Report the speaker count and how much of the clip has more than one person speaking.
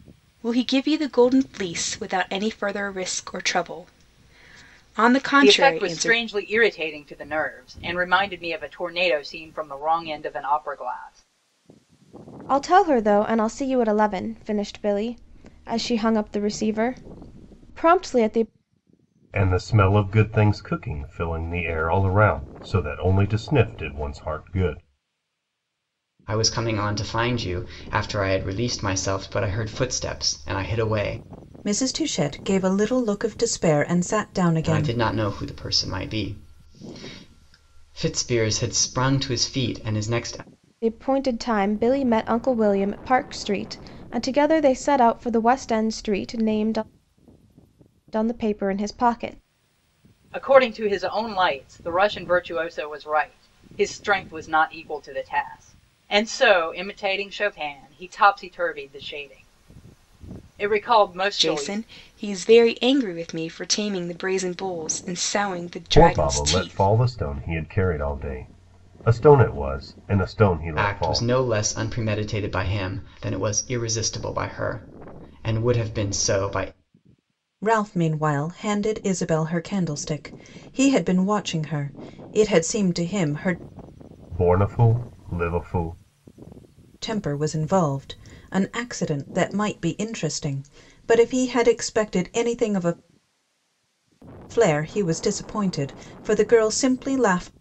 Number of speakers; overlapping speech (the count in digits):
6, about 4%